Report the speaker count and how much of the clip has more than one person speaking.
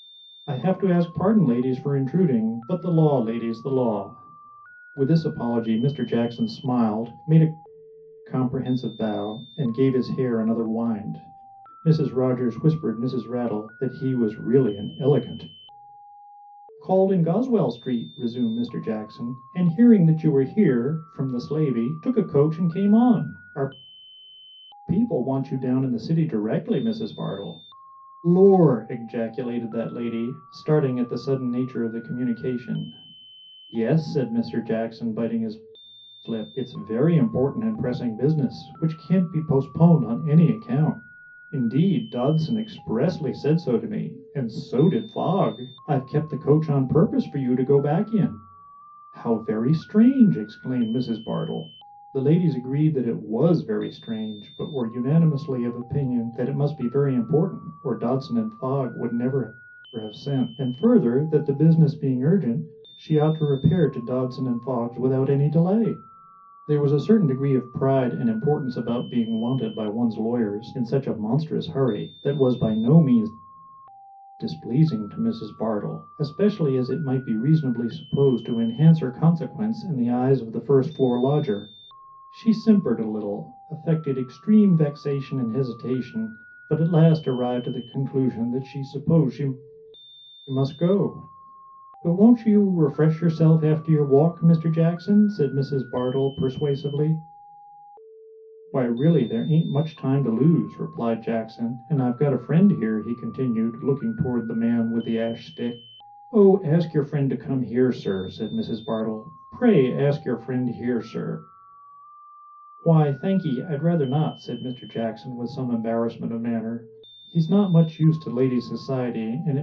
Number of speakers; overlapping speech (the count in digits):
1, no overlap